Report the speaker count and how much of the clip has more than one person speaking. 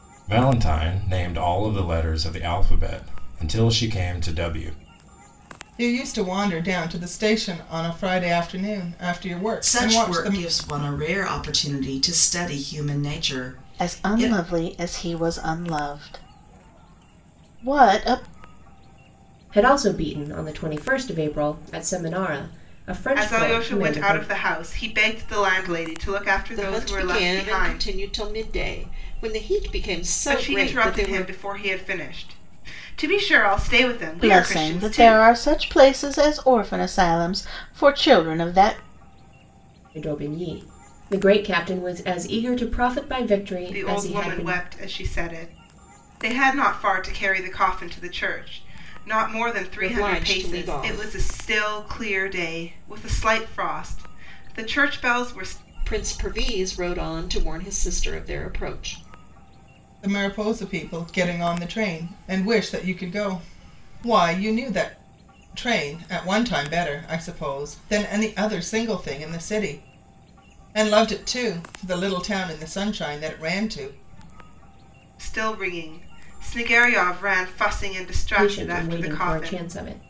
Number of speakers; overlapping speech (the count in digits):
7, about 12%